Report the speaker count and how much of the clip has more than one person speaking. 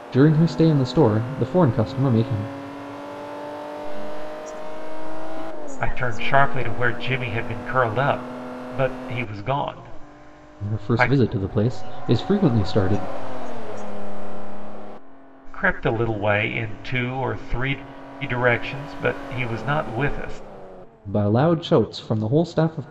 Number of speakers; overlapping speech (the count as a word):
three, about 10%